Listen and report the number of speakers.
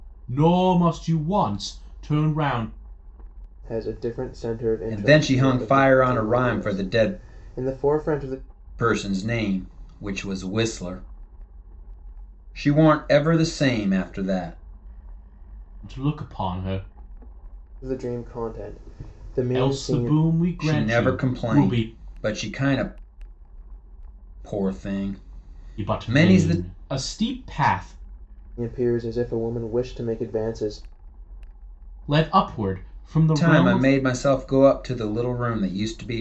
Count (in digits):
3